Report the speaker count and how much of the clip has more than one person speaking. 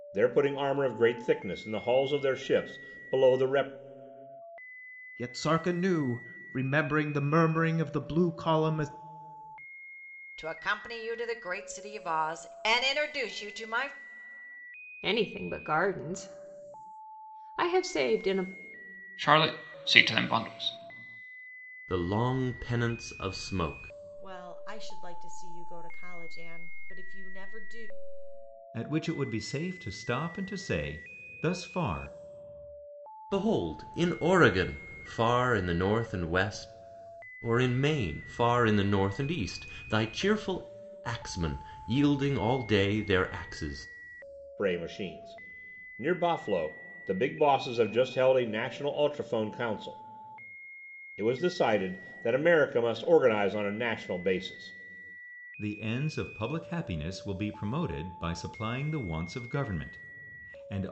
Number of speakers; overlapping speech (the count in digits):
8, no overlap